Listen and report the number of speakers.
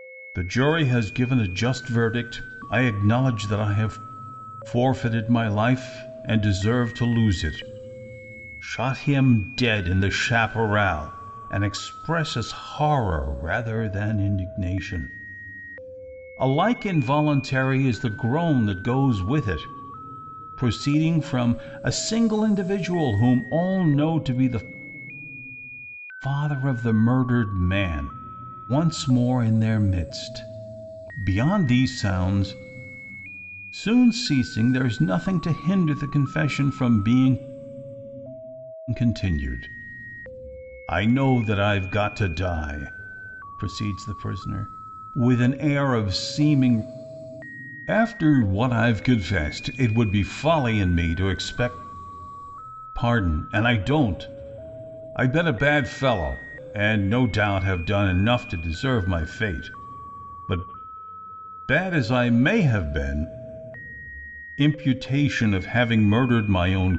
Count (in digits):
1